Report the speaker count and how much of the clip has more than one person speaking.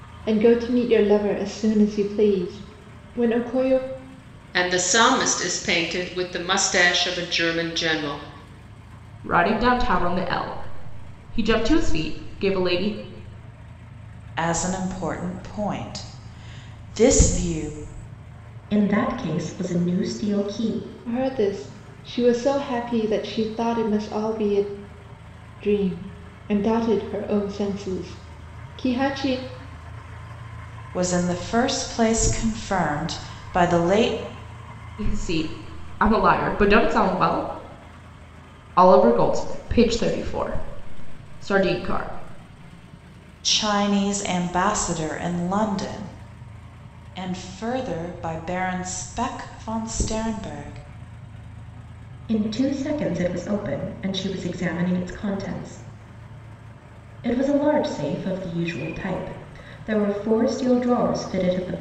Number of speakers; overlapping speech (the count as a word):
five, no overlap